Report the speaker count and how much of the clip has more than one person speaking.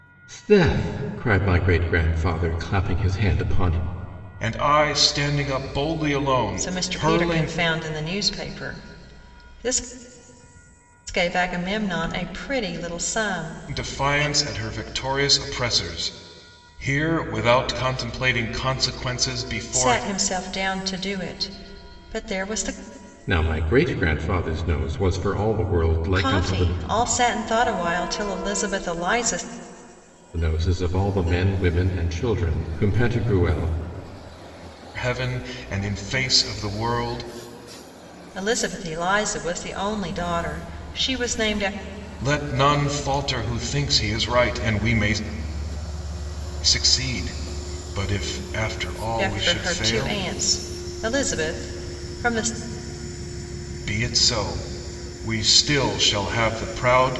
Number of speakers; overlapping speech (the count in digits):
3, about 6%